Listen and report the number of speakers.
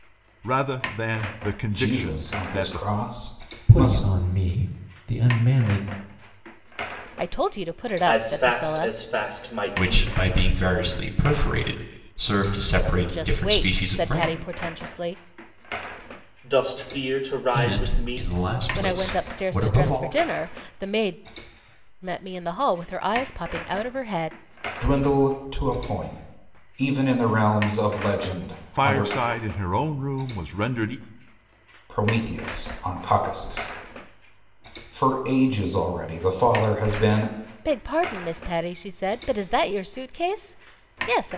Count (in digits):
6